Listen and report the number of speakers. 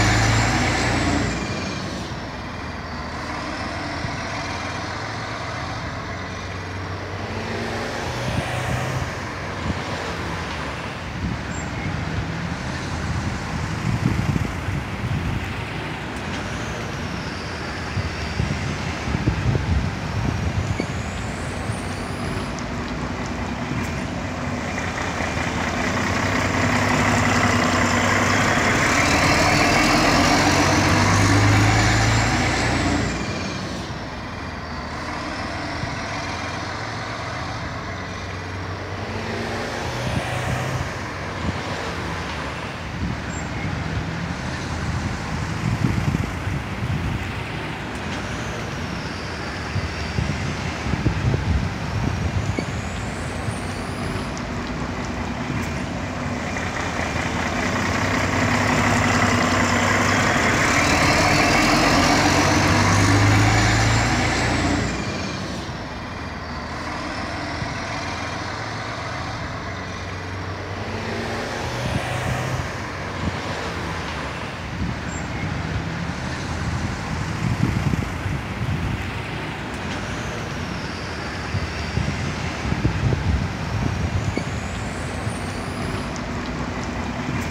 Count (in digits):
0